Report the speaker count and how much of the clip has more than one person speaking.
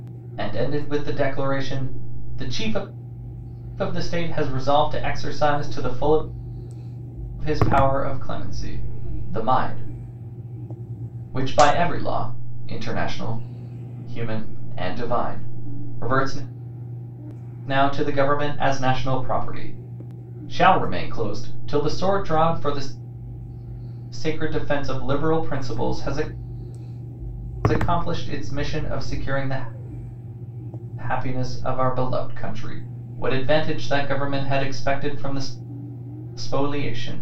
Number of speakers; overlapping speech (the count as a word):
one, no overlap